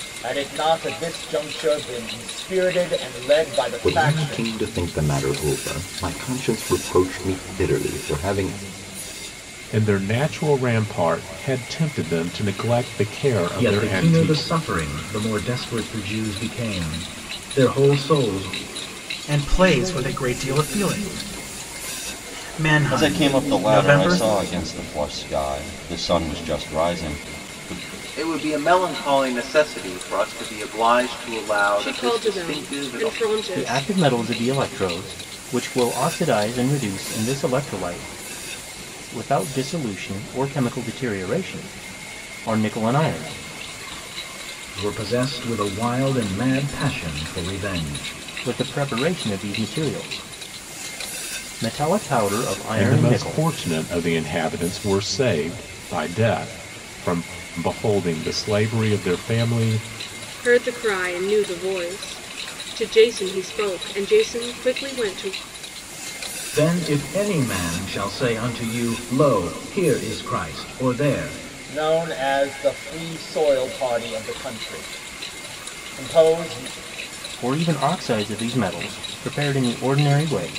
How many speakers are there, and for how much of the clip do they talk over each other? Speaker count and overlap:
9, about 7%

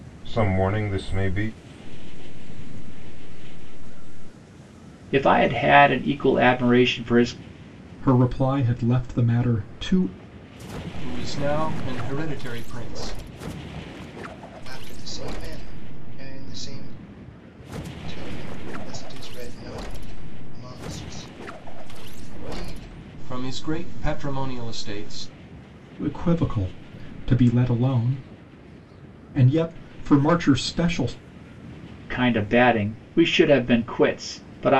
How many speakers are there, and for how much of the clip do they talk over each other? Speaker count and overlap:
6, about 4%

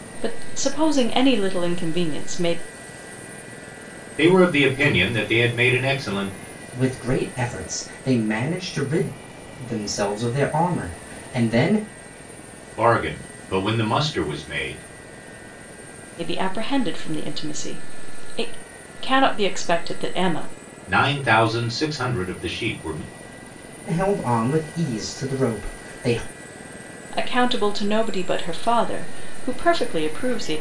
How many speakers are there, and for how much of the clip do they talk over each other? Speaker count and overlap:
3, no overlap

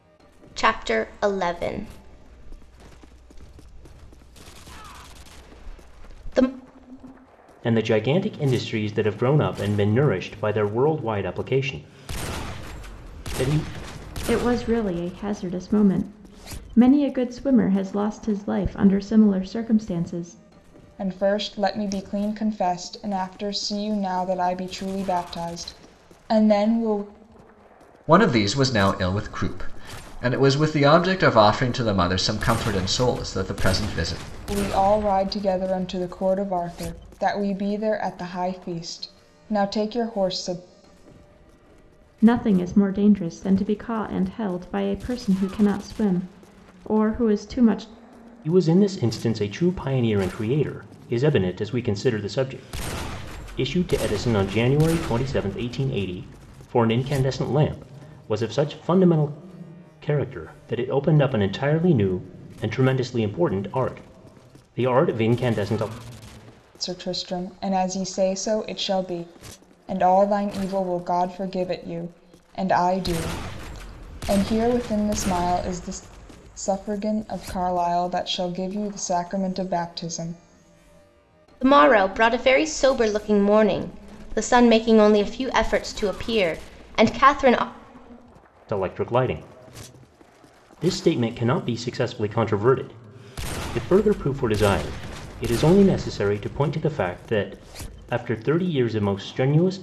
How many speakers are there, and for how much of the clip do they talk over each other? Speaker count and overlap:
5, no overlap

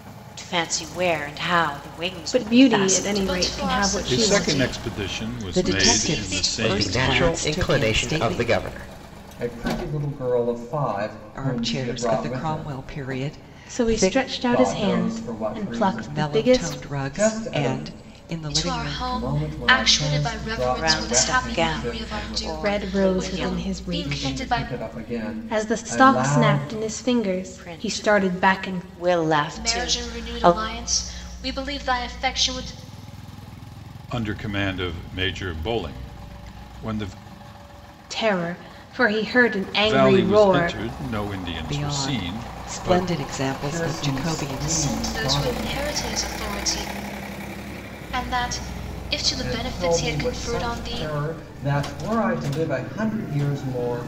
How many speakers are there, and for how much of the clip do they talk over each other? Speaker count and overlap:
7, about 52%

